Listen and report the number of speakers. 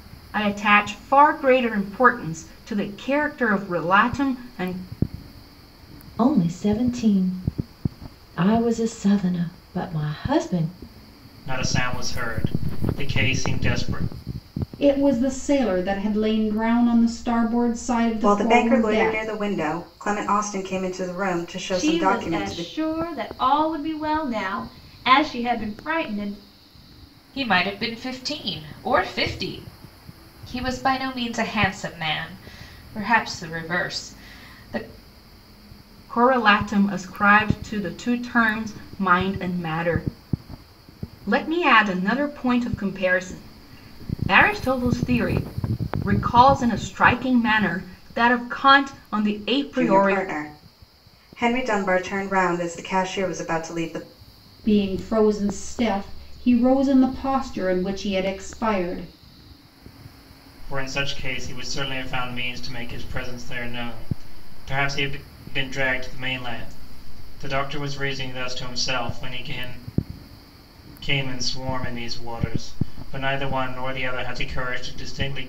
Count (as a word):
seven